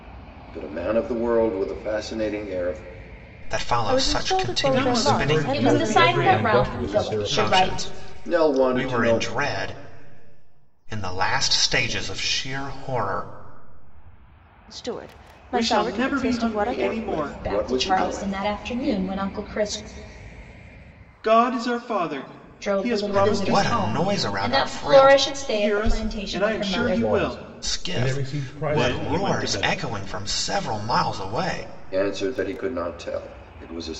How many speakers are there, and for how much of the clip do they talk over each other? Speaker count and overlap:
6, about 46%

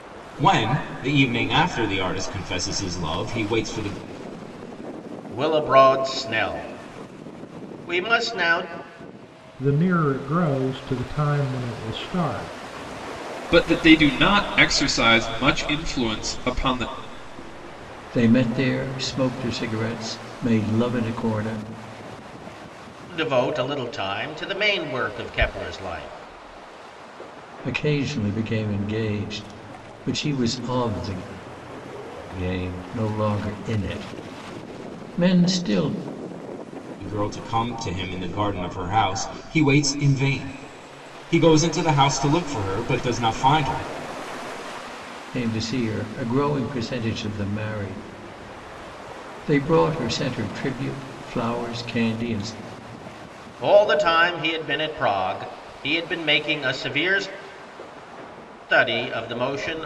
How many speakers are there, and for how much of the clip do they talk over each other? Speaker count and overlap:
5, no overlap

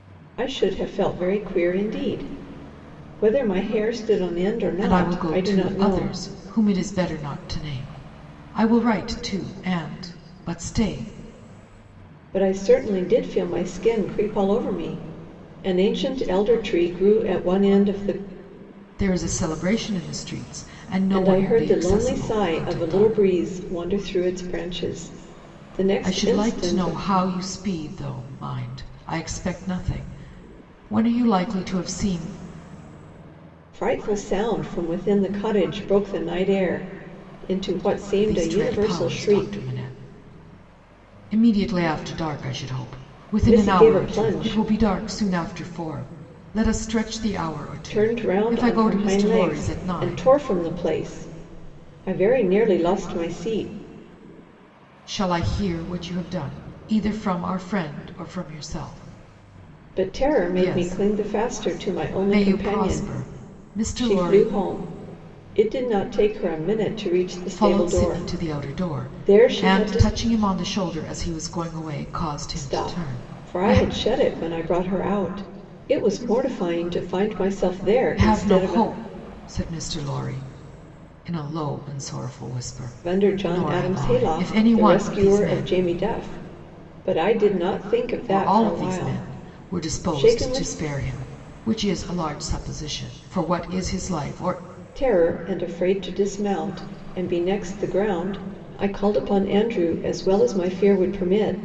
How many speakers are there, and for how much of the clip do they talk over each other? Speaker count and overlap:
2, about 22%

